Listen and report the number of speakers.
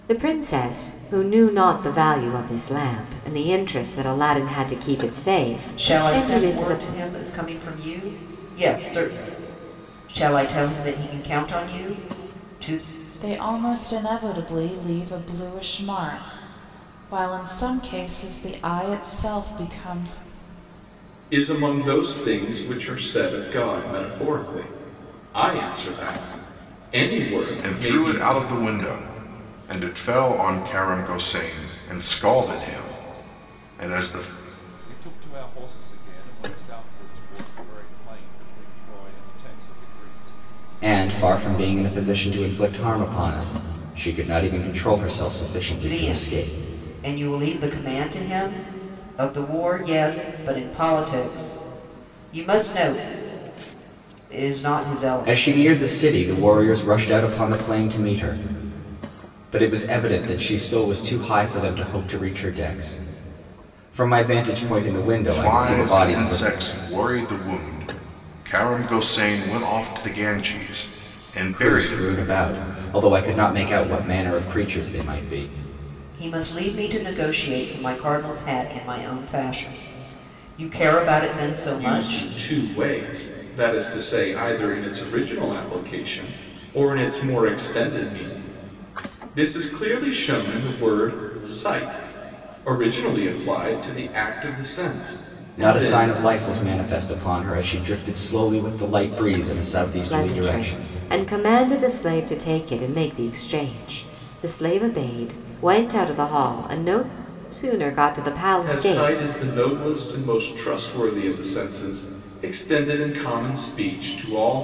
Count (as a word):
seven